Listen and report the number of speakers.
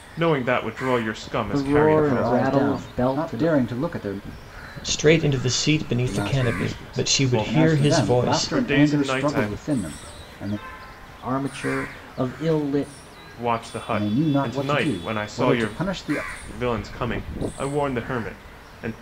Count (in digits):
4